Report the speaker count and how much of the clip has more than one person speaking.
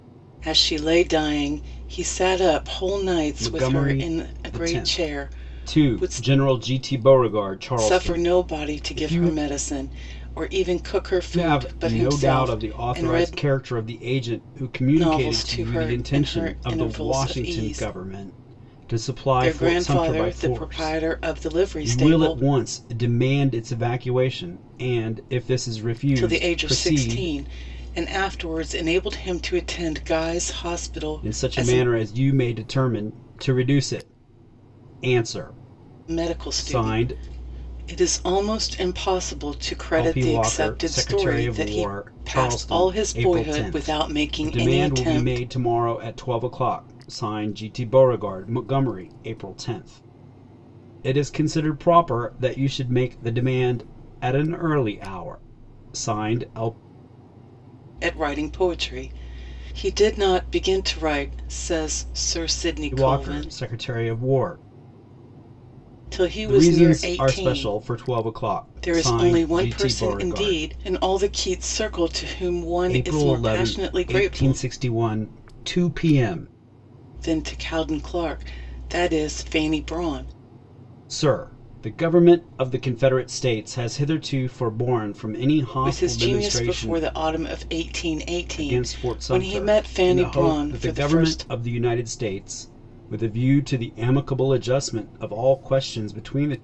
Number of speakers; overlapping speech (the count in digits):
2, about 30%